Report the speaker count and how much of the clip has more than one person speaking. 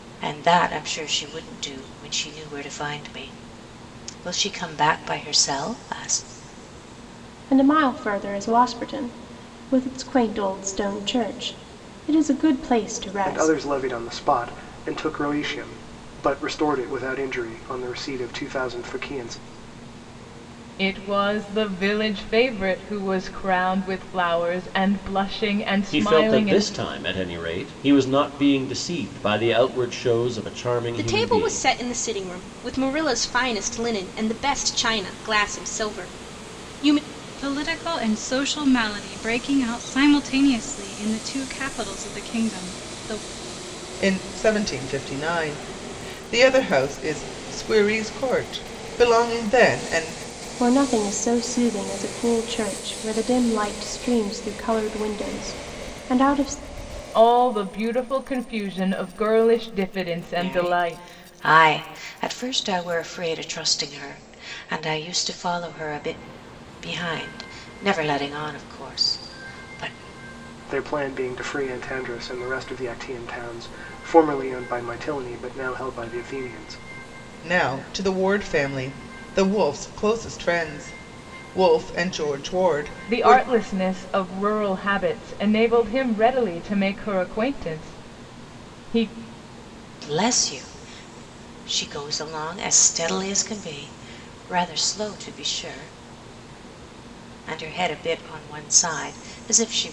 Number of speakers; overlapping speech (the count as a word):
eight, about 3%